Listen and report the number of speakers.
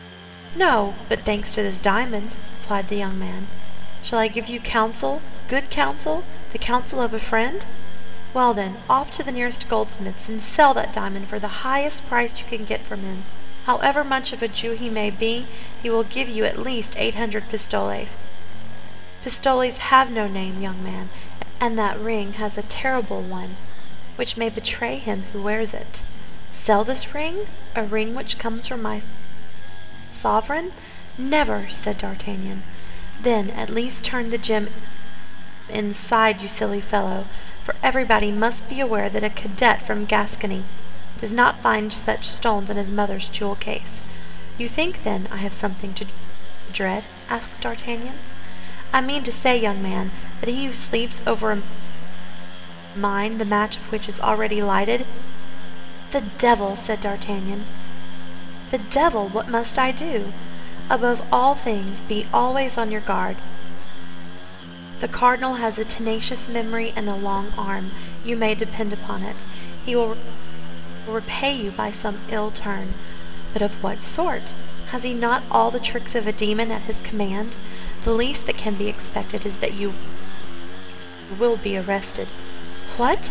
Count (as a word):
one